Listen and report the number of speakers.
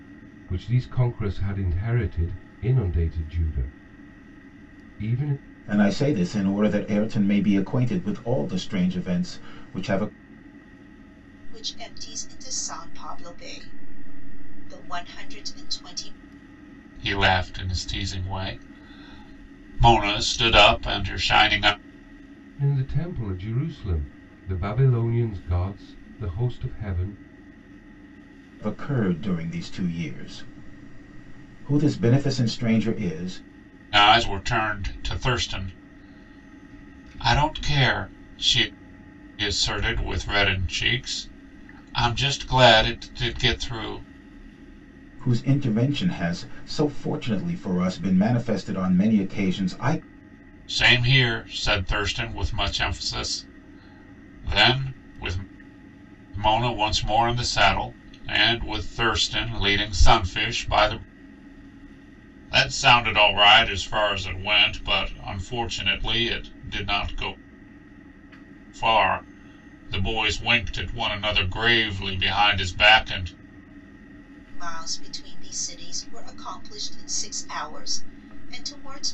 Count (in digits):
4